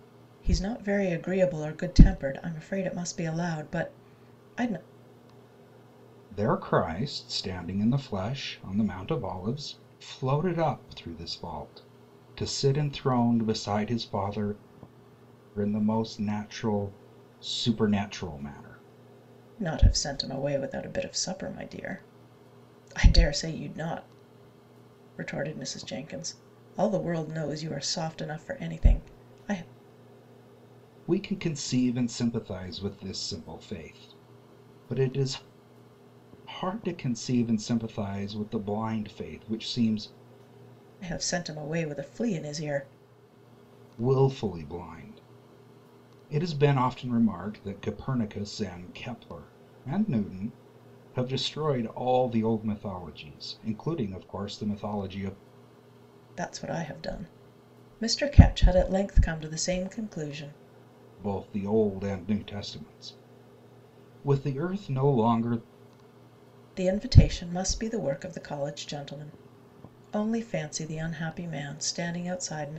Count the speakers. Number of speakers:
two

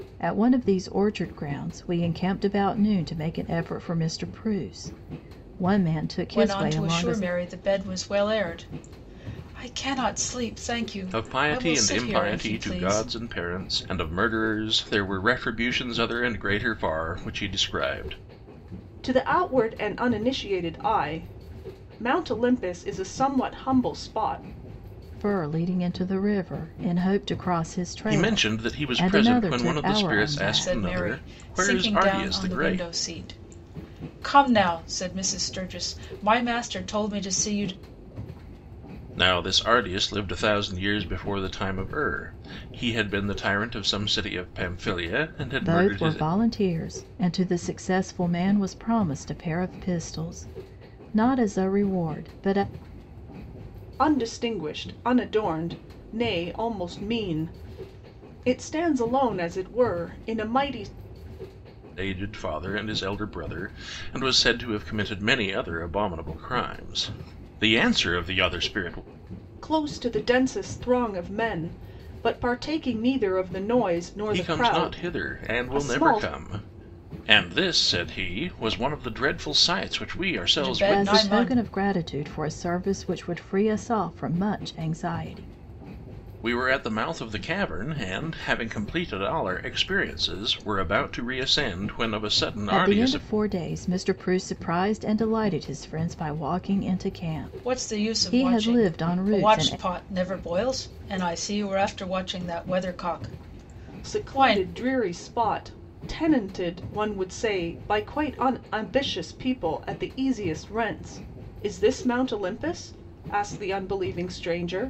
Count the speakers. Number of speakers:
four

